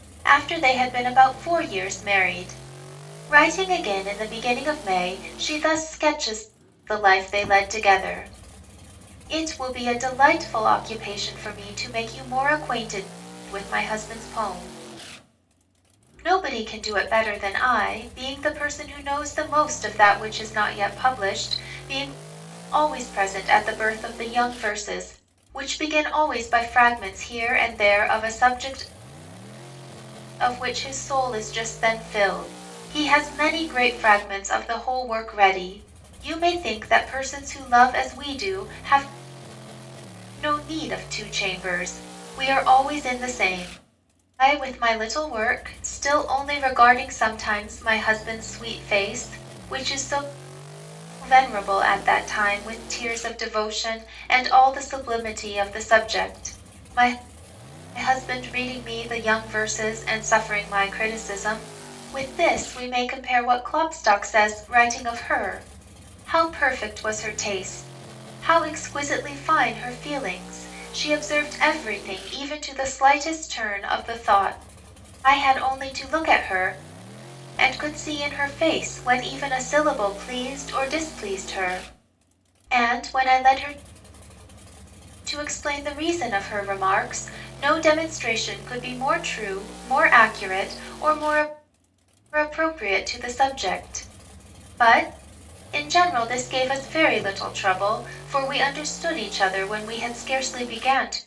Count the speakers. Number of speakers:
1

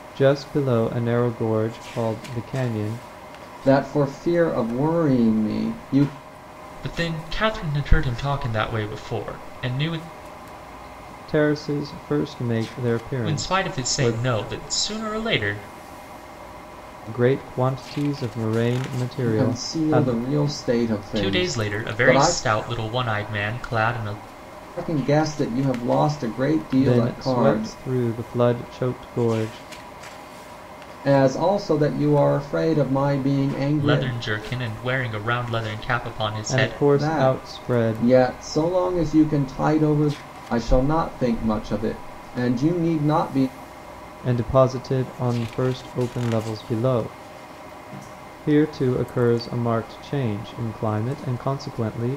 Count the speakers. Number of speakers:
3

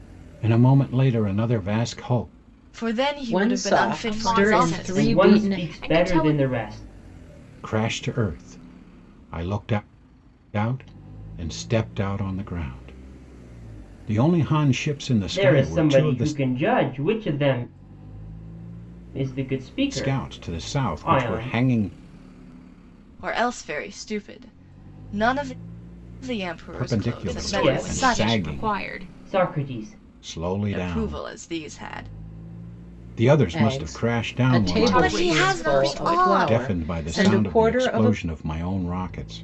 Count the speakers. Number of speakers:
5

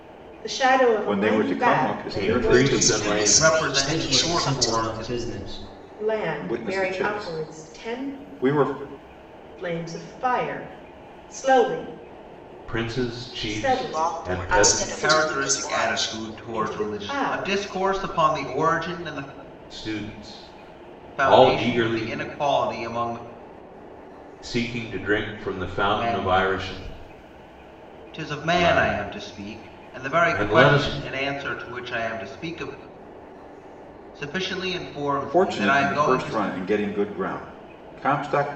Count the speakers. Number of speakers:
6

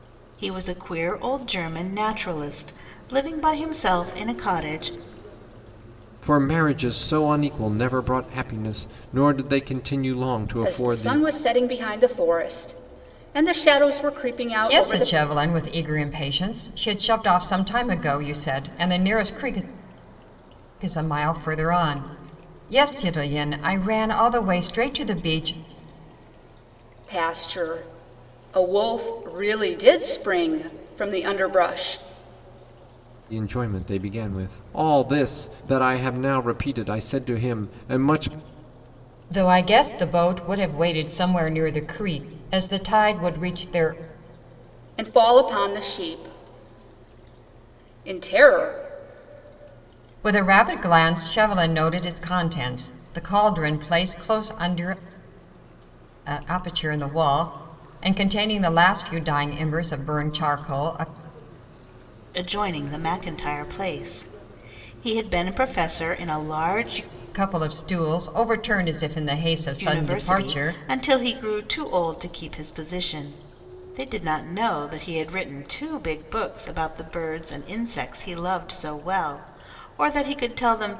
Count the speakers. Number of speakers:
4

